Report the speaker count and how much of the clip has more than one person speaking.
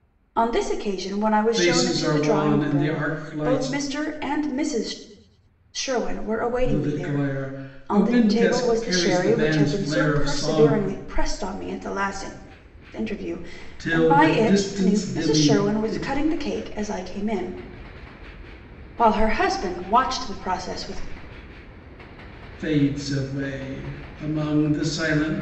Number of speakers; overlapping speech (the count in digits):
2, about 35%